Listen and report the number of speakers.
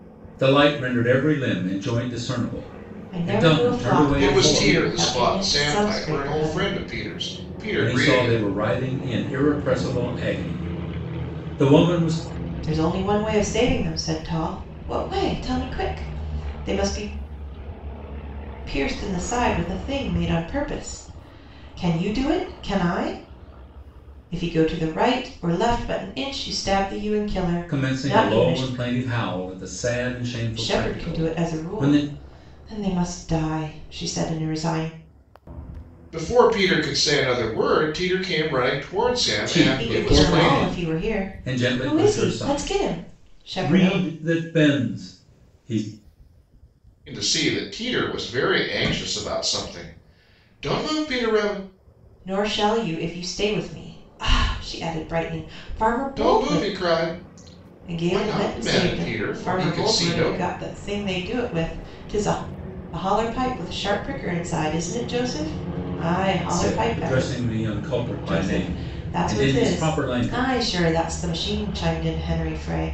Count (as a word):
three